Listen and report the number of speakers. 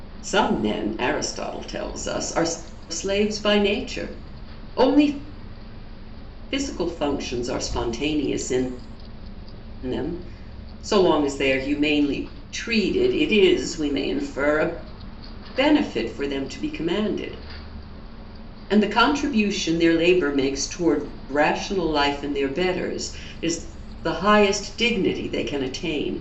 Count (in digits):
1